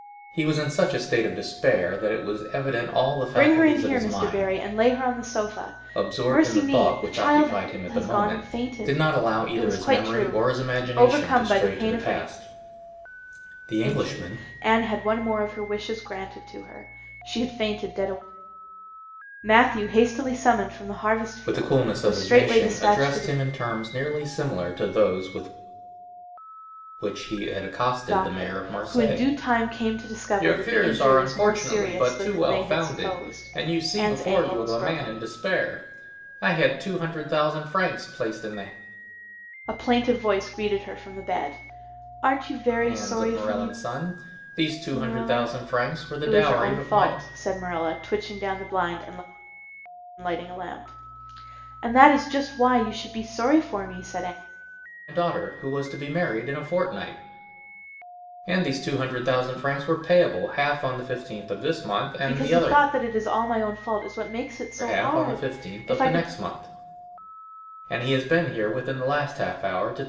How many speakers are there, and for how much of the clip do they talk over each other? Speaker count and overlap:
2, about 31%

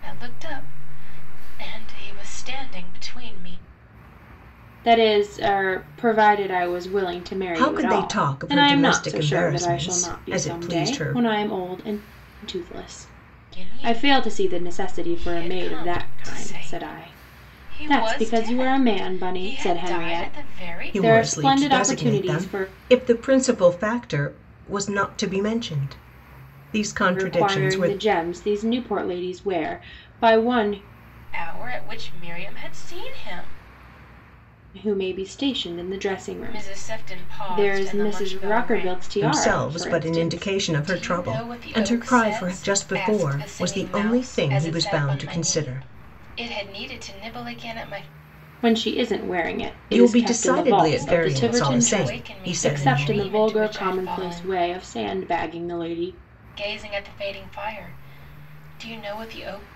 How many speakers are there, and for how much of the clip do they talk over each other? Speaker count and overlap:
3, about 44%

